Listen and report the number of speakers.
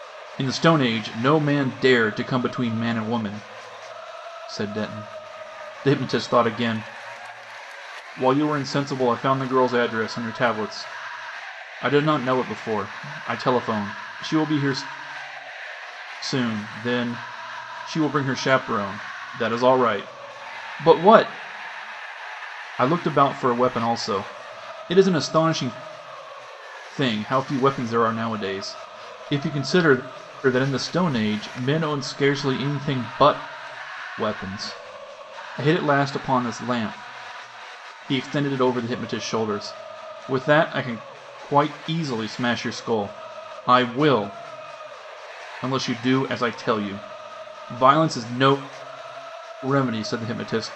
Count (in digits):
1